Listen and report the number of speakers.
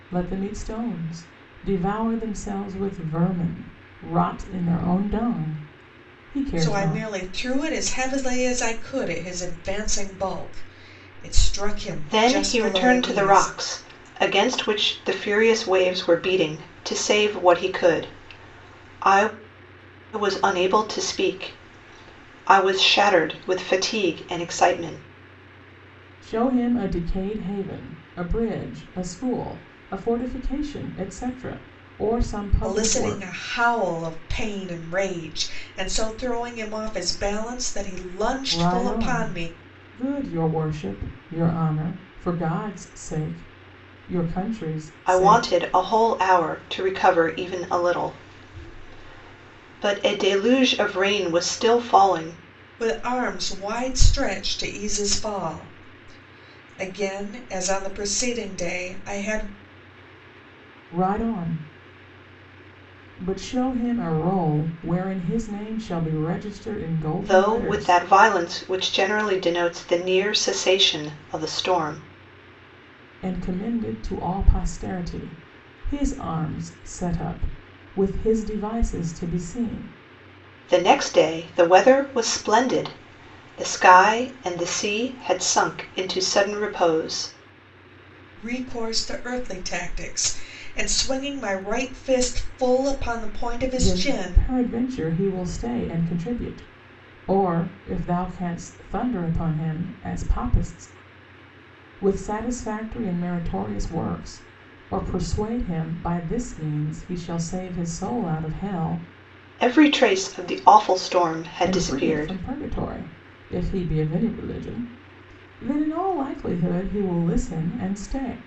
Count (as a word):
three